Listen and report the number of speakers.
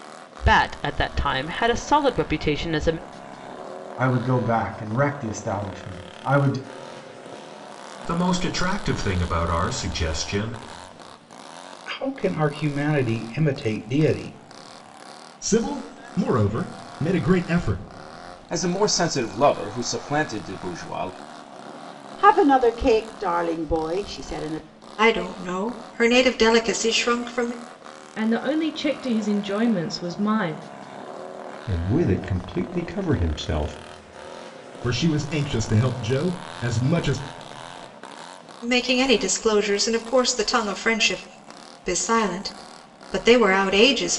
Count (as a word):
ten